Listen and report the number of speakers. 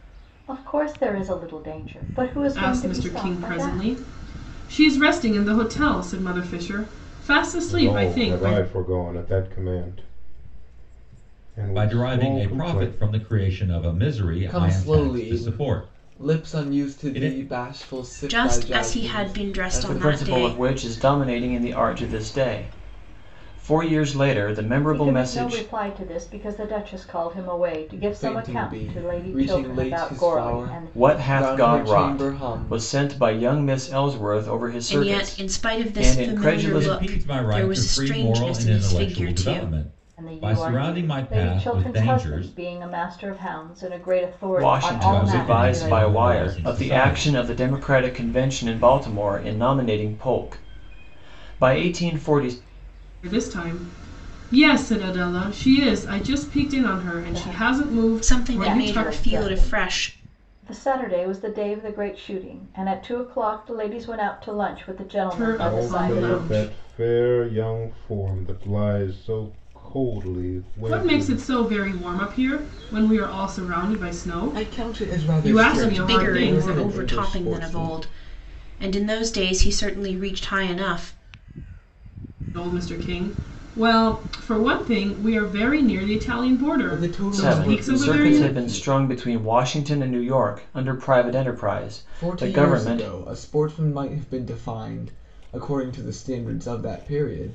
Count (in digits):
7